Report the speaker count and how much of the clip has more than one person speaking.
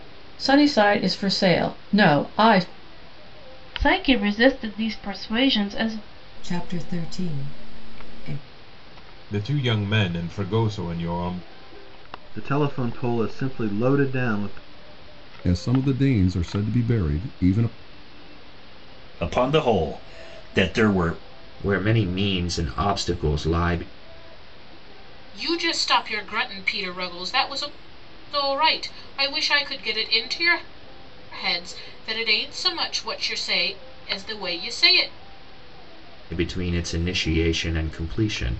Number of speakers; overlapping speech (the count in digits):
9, no overlap